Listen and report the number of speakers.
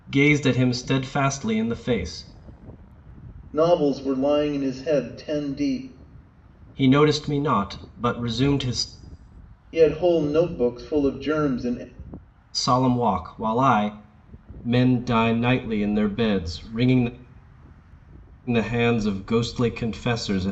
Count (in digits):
2